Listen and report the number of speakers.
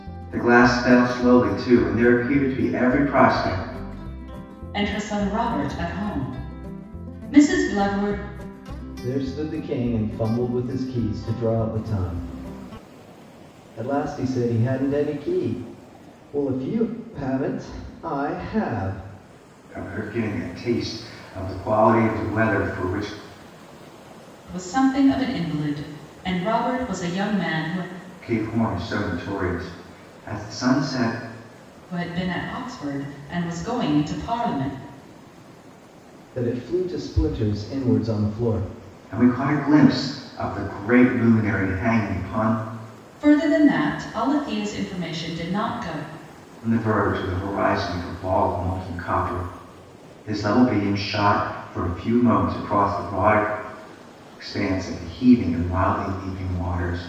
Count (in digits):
3